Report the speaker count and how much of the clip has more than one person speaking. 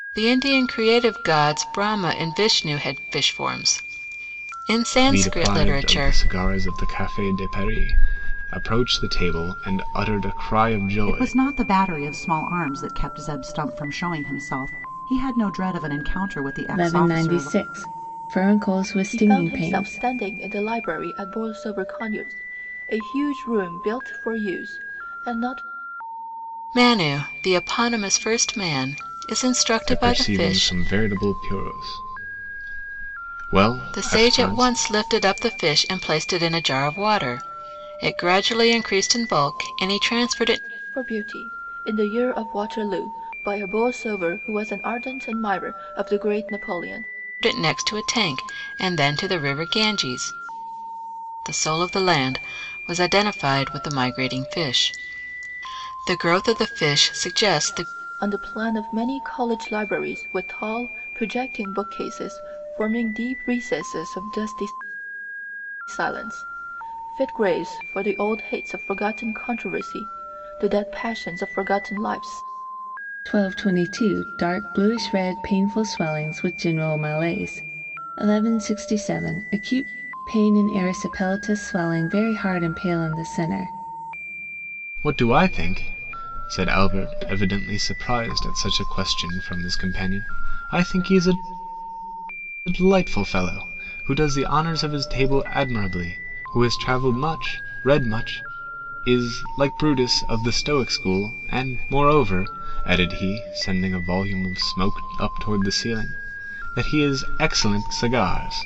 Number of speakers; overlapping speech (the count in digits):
5, about 5%